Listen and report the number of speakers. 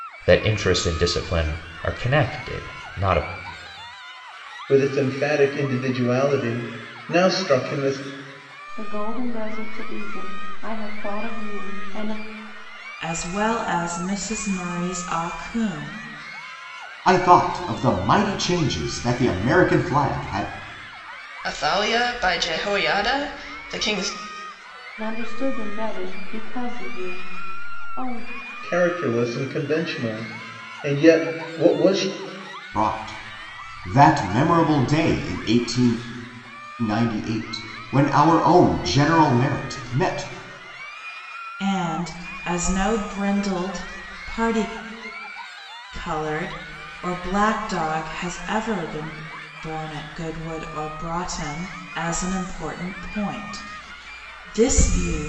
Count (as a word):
six